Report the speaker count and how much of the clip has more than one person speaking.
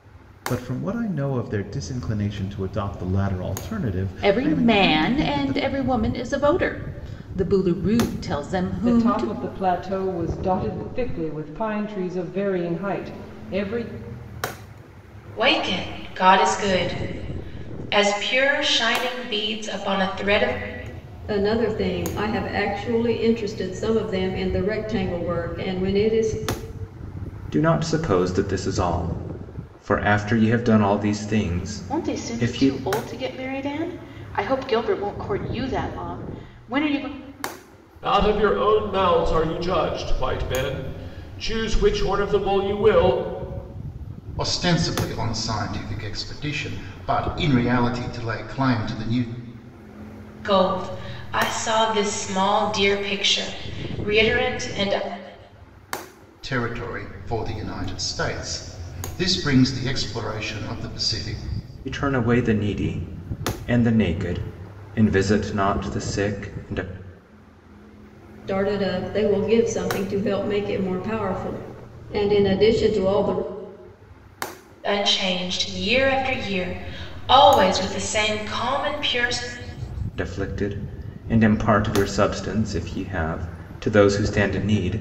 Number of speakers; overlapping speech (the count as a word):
nine, about 4%